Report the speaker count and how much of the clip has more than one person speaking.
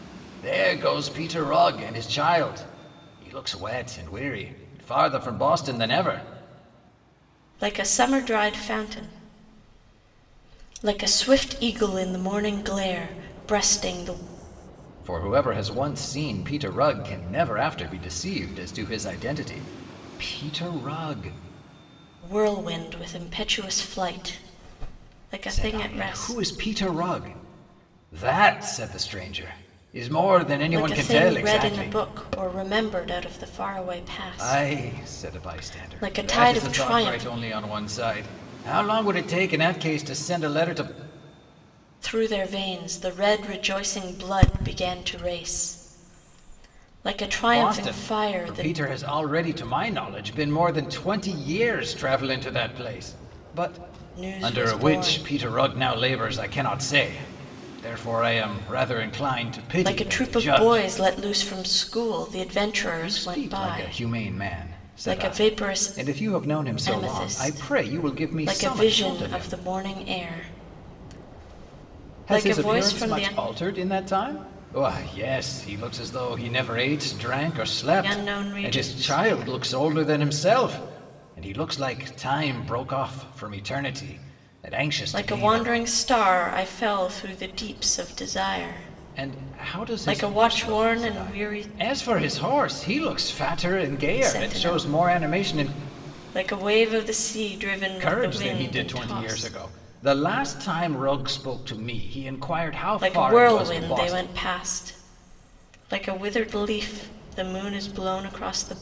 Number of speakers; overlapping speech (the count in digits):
2, about 22%